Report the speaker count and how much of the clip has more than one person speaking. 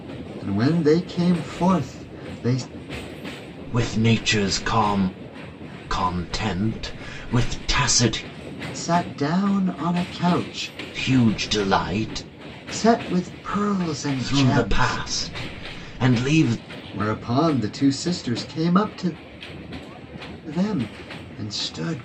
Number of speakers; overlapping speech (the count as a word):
two, about 4%